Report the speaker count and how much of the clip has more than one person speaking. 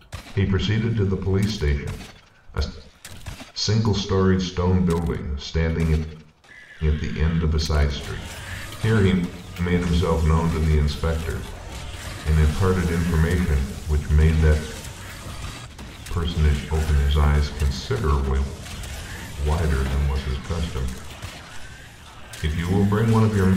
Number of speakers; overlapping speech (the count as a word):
one, no overlap